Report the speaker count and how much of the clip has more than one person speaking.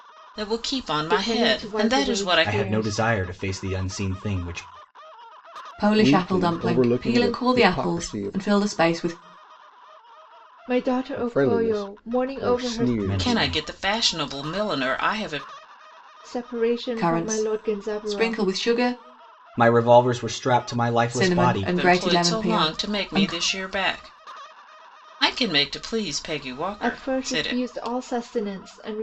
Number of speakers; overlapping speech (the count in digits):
5, about 39%